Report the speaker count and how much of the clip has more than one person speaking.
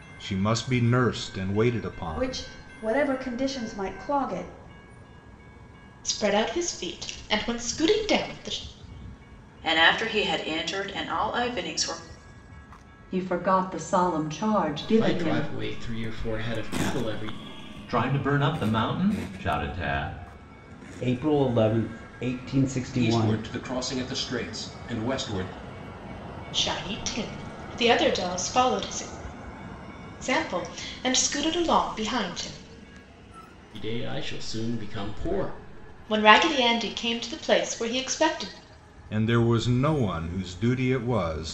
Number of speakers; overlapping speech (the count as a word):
nine, about 3%